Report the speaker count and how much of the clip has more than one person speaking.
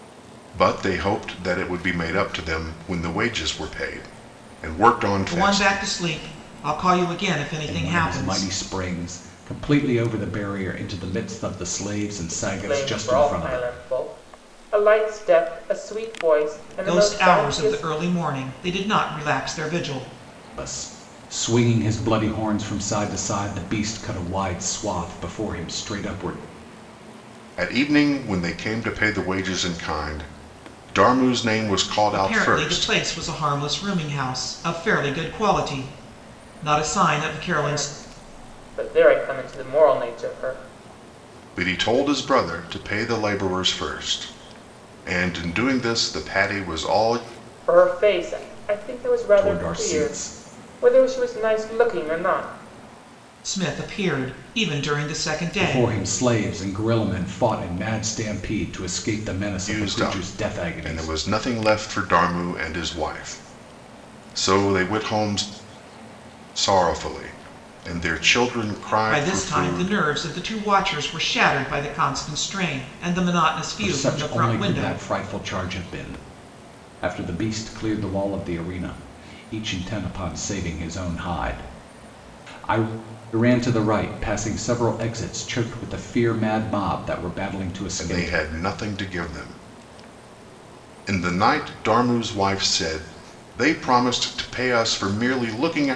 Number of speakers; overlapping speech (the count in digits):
4, about 11%